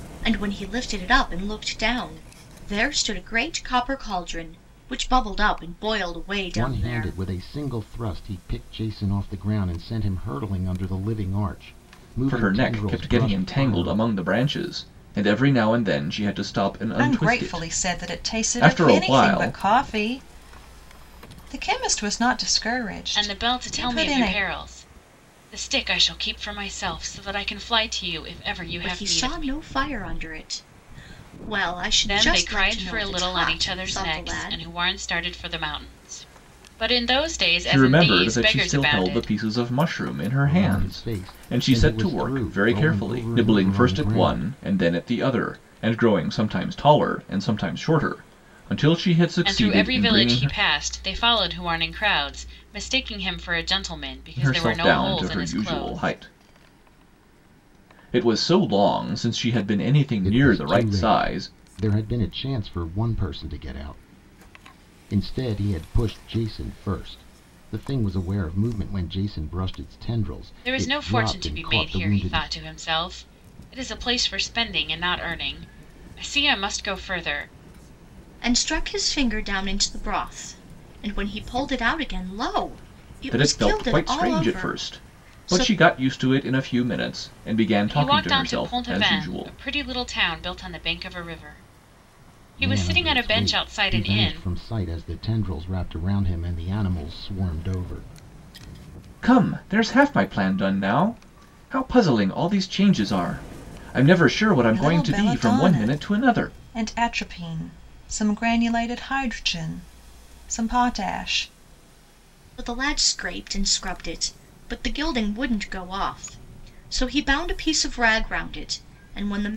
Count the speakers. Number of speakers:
five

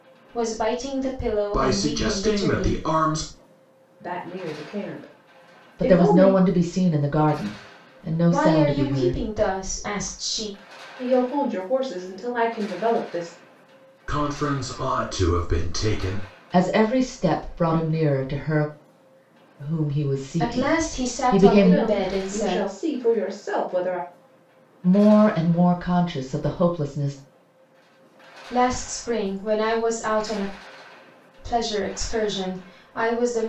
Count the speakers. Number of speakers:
four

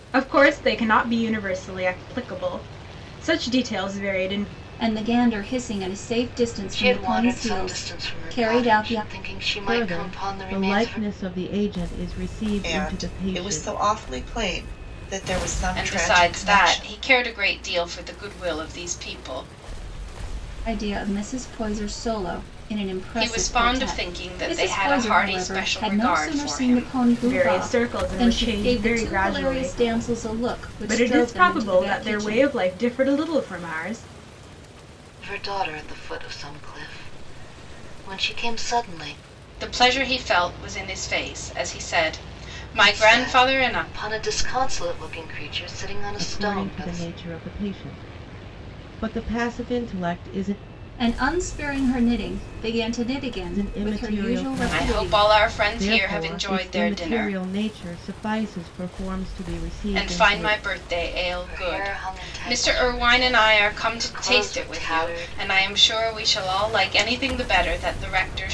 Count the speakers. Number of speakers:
six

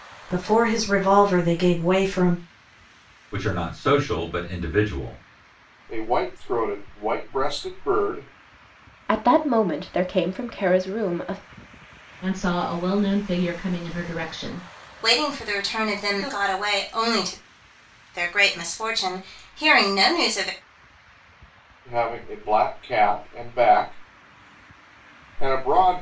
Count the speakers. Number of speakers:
six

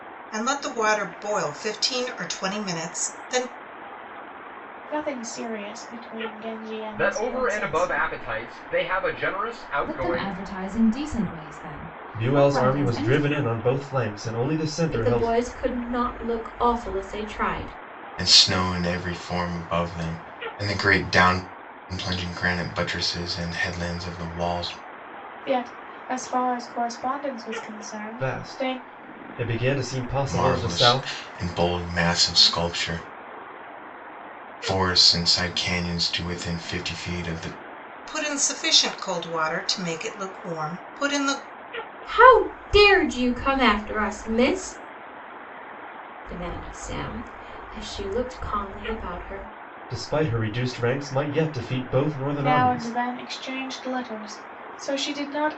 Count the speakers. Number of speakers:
seven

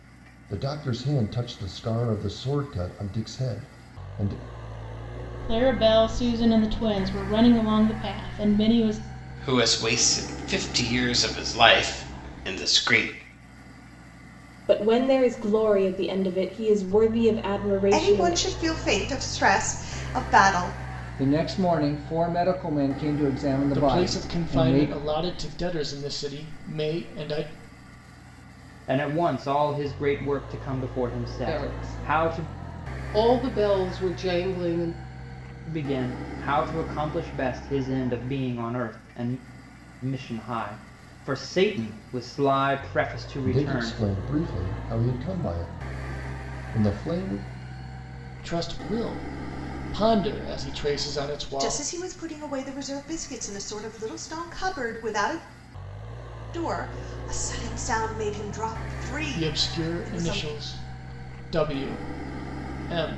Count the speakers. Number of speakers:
nine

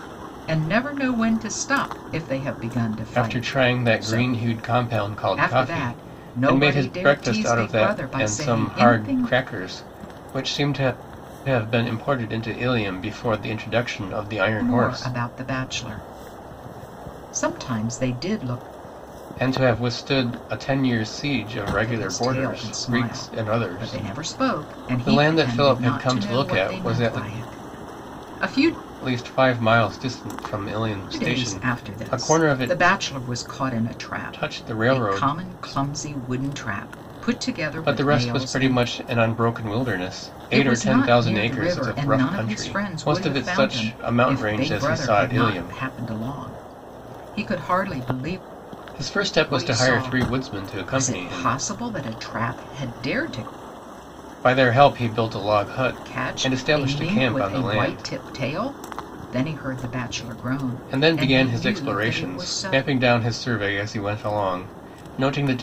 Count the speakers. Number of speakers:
two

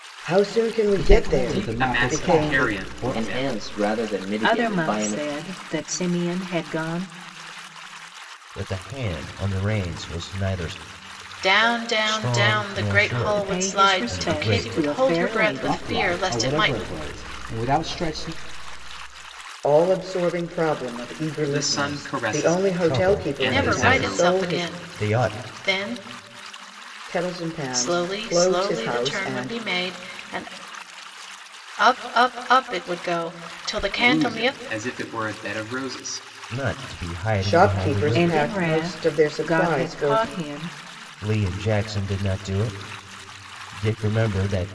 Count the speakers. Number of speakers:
seven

